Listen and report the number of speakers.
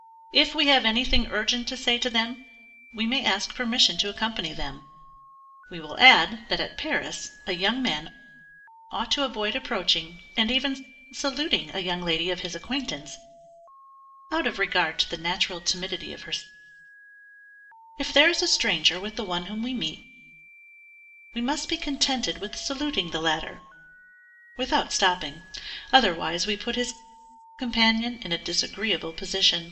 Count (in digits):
1